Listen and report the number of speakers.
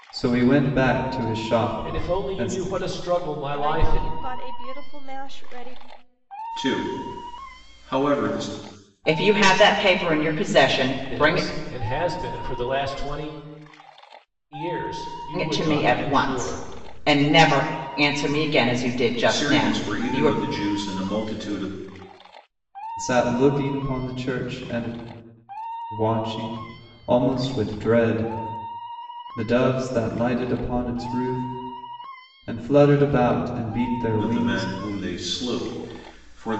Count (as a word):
five